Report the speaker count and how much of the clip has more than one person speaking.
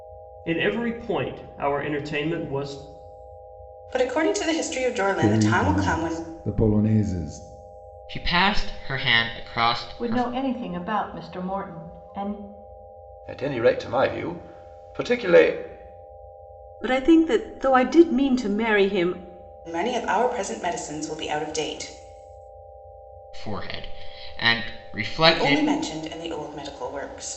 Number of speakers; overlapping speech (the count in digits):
7, about 7%